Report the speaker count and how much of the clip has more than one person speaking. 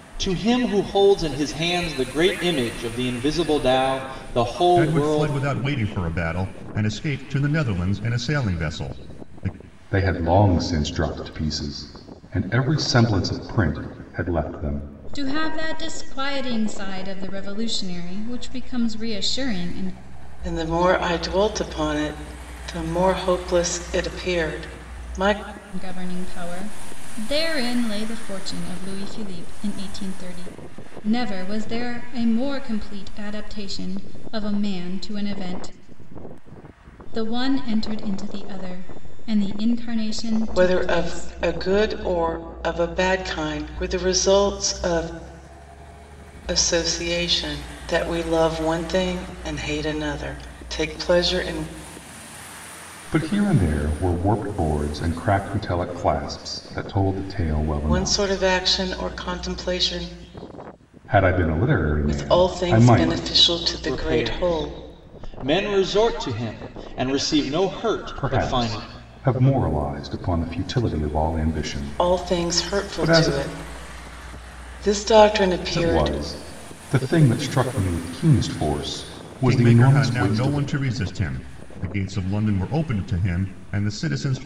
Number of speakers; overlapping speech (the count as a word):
five, about 9%